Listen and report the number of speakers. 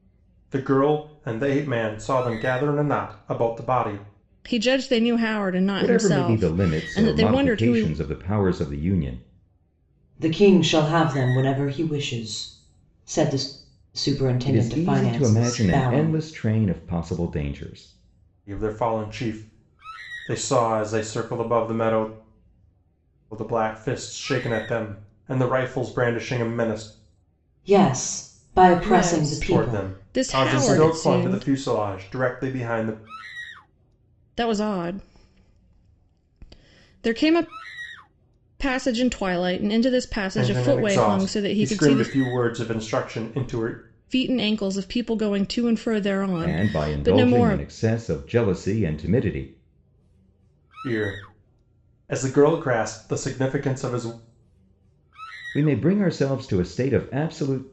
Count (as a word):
four